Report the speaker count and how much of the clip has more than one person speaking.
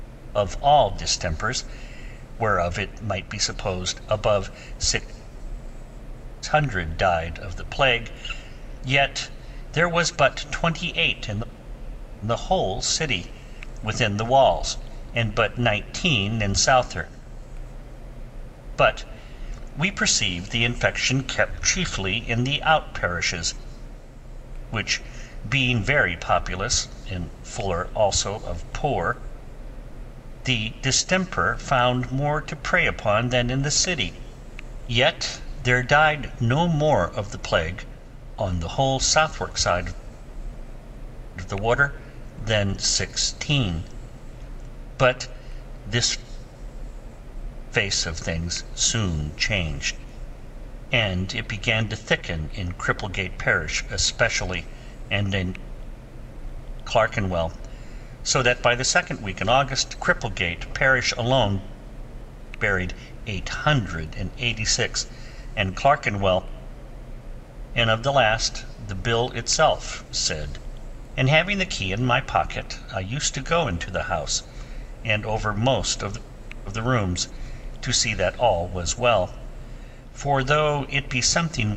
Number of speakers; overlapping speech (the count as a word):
one, no overlap